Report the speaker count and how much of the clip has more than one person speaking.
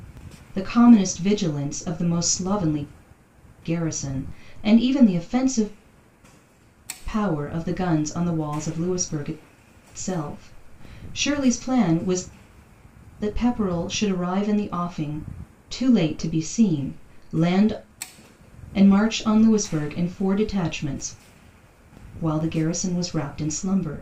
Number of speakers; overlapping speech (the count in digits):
1, no overlap